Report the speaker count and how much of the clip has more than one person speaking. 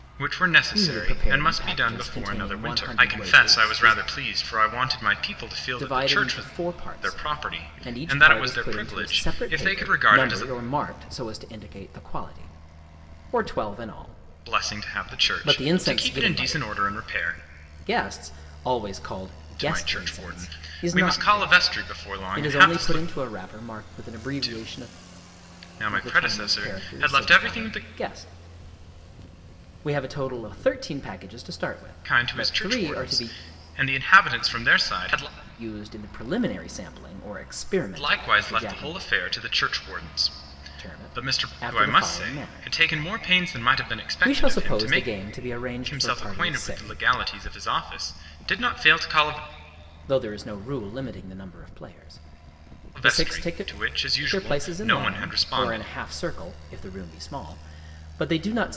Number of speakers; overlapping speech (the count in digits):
2, about 43%